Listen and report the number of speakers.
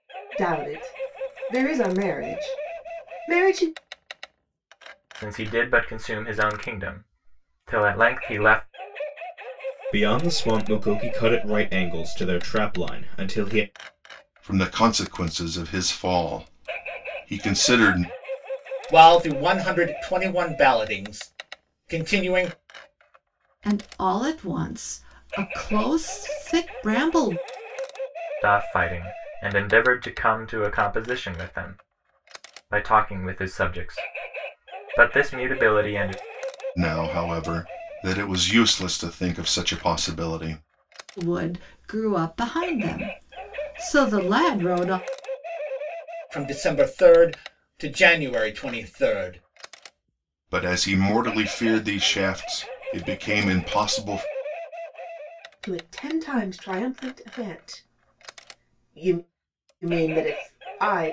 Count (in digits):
6